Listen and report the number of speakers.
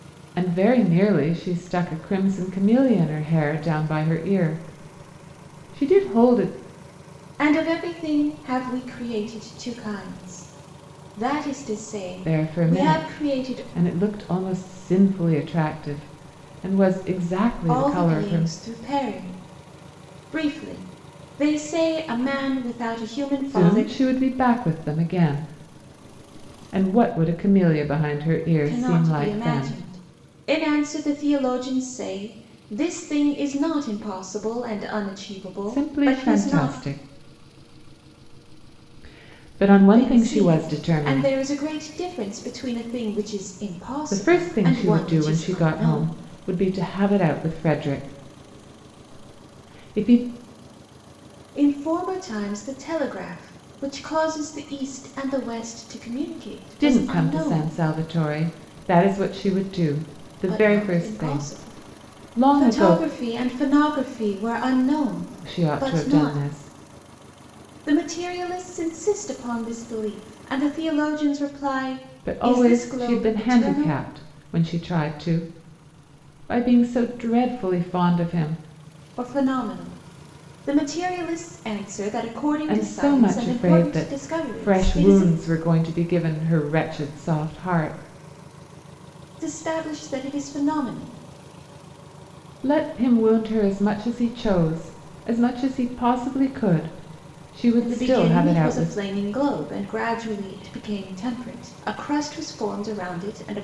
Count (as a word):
two